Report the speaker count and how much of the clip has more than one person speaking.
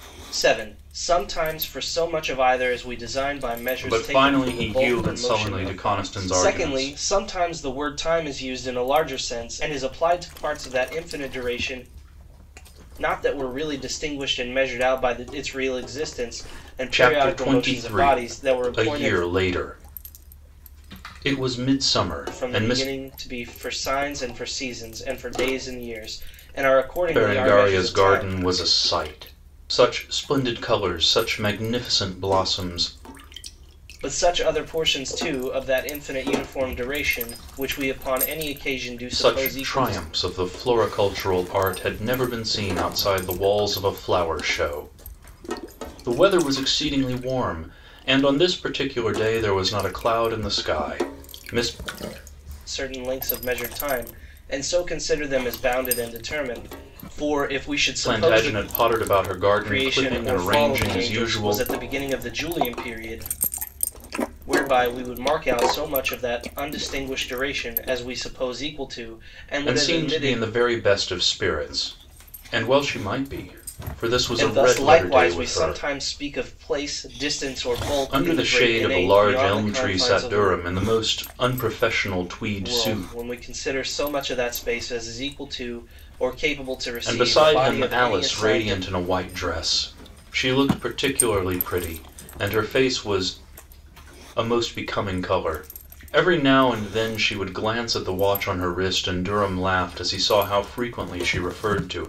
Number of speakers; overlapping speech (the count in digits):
2, about 18%